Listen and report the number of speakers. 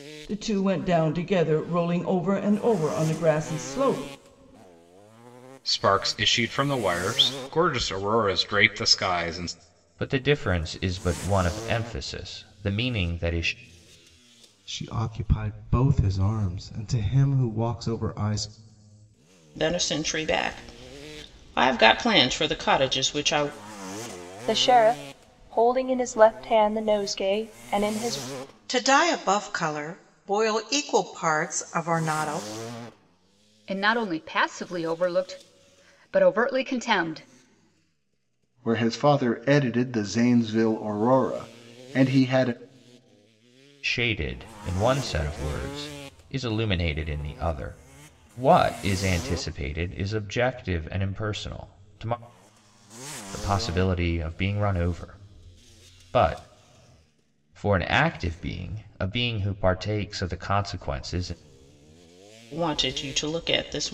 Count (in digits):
9